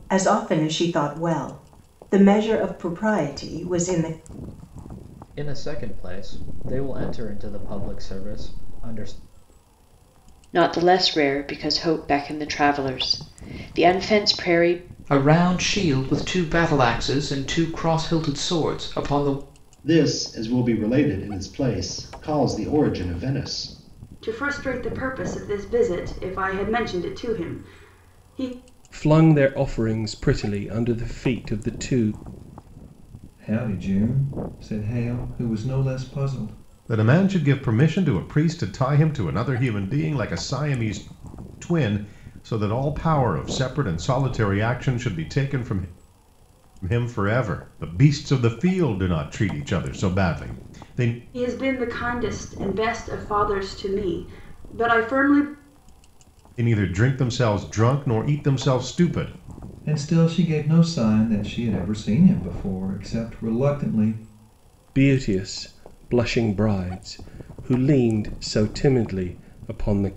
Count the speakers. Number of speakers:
nine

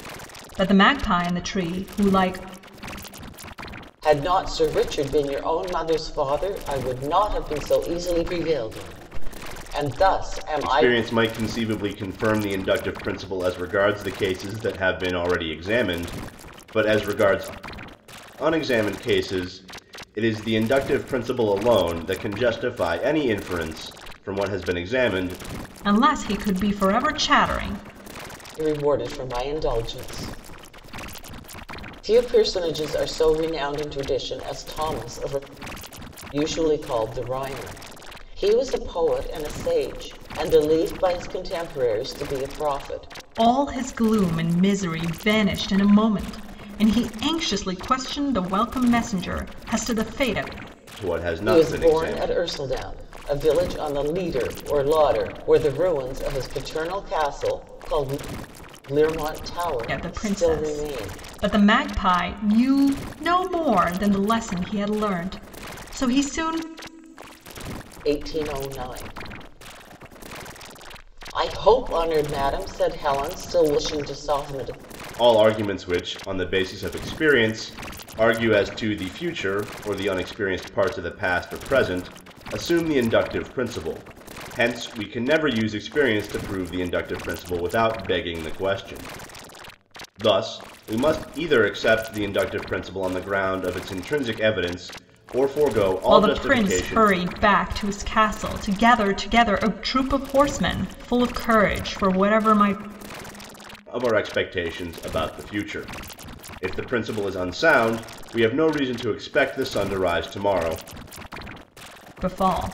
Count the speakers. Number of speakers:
three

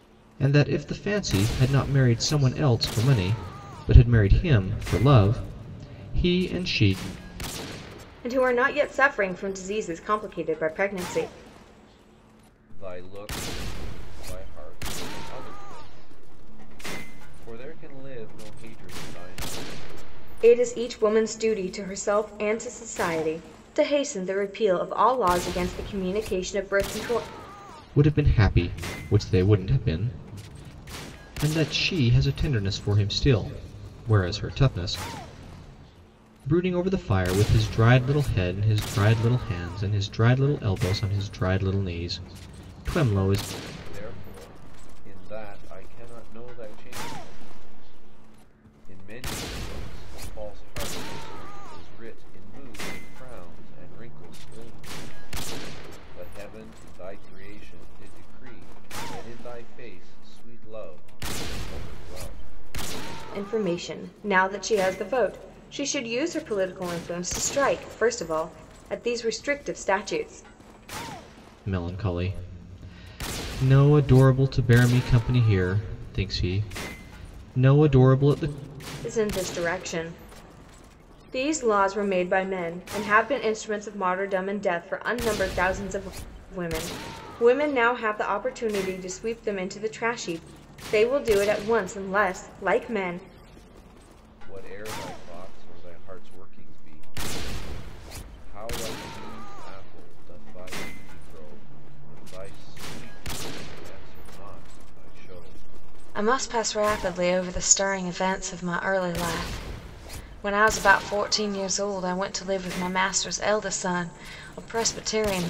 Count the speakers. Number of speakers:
three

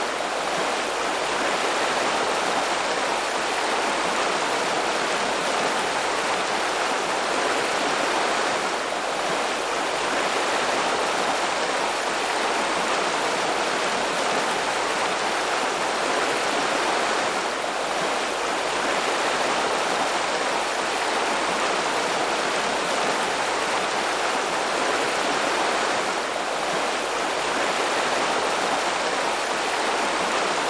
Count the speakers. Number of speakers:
zero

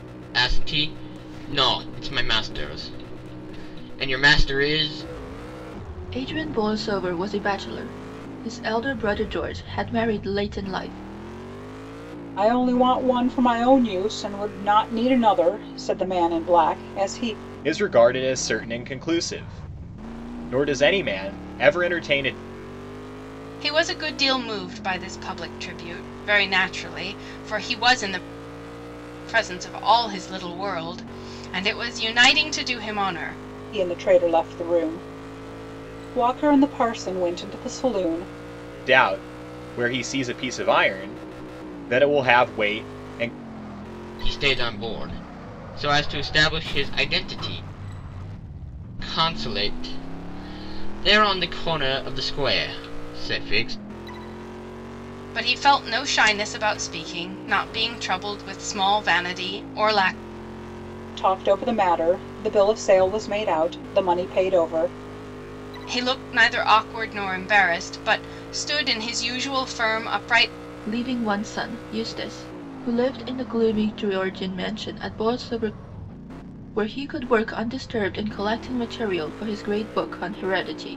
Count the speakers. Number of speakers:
five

